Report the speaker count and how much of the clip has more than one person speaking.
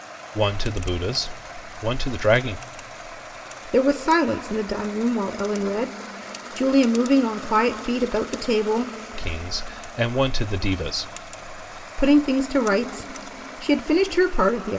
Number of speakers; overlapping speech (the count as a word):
two, no overlap